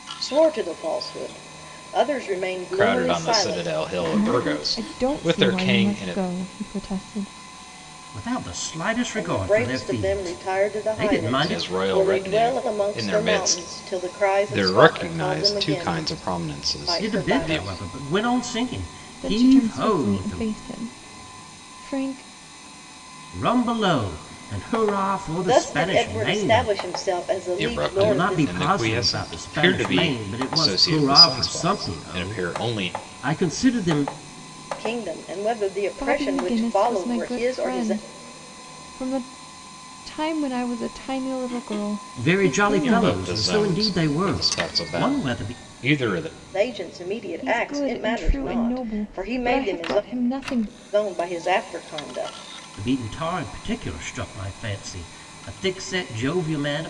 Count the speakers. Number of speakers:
4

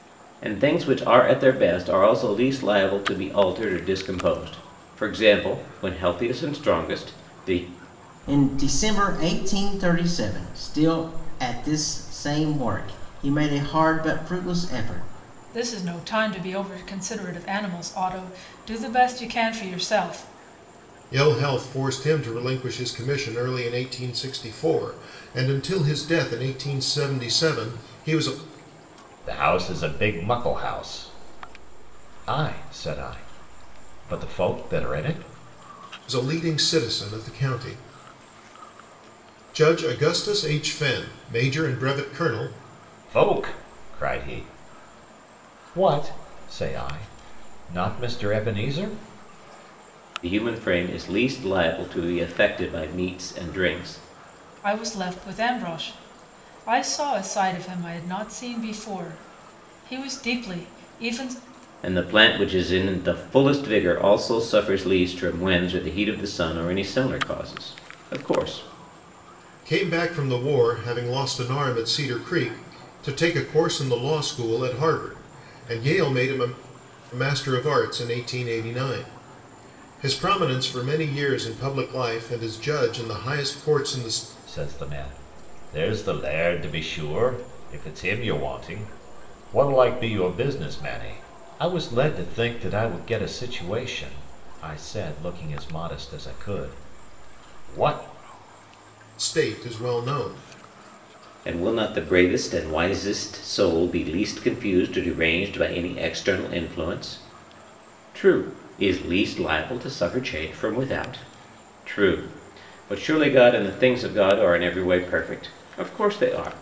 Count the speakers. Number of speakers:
5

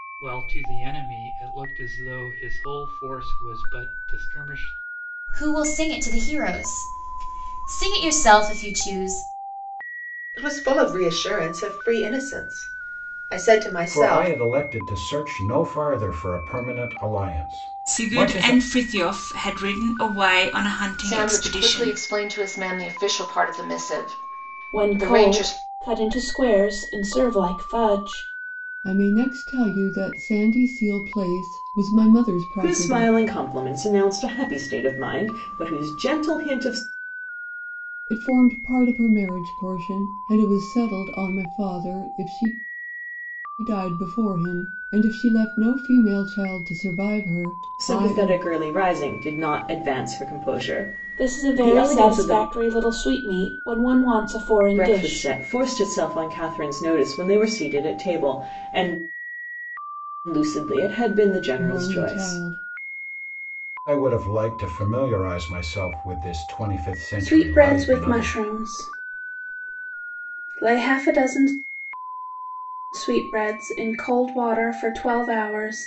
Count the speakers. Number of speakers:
9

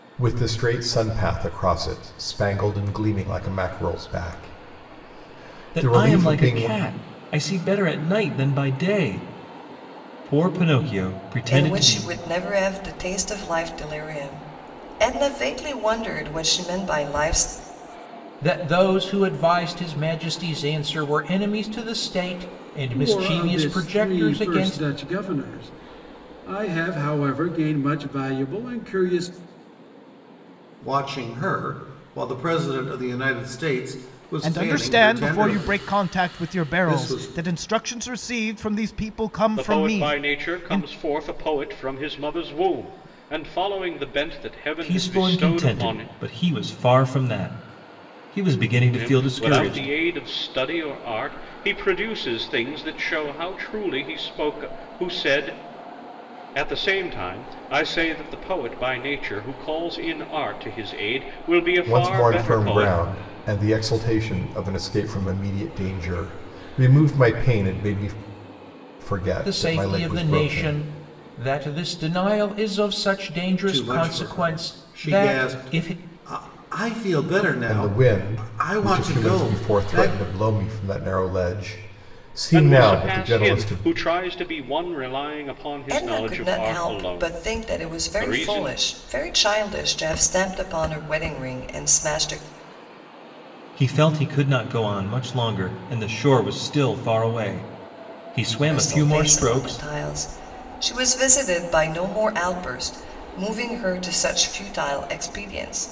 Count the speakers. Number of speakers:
8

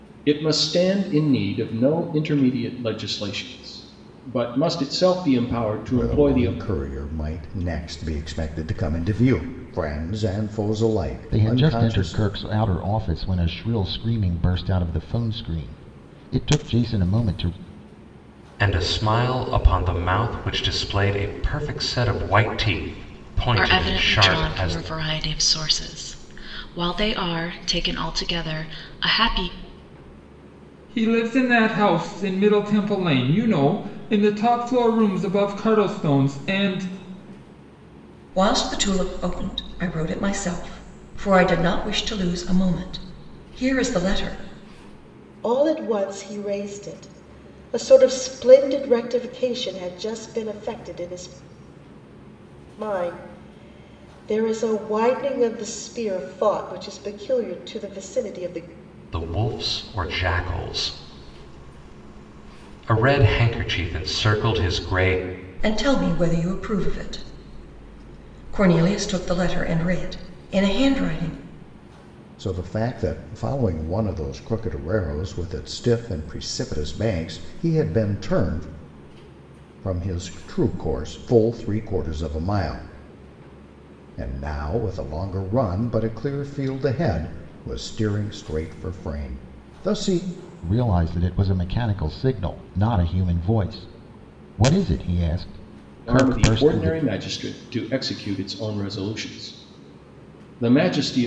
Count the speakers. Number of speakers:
8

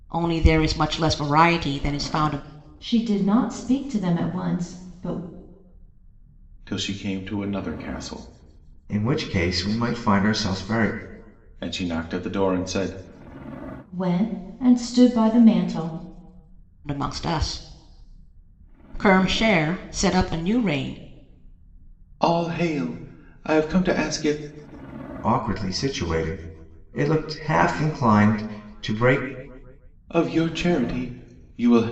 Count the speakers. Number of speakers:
4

